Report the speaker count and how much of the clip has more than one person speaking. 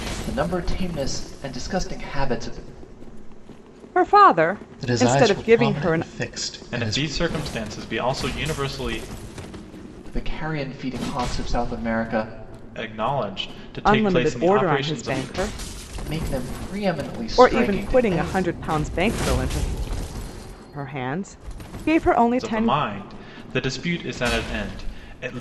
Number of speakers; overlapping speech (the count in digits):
4, about 18%